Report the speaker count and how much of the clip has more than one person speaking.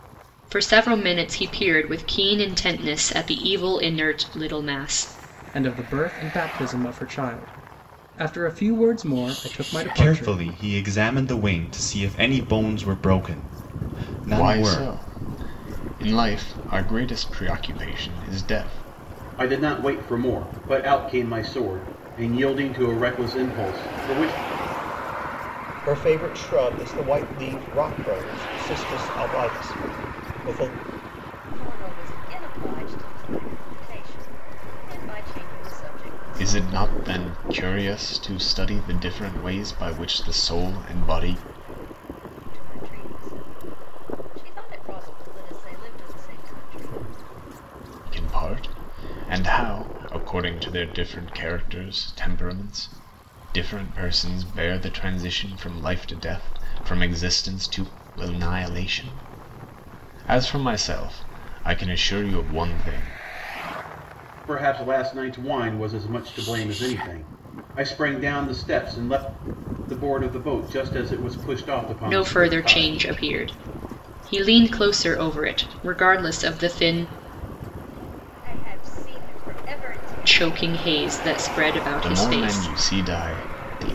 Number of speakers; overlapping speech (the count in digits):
7, about 4%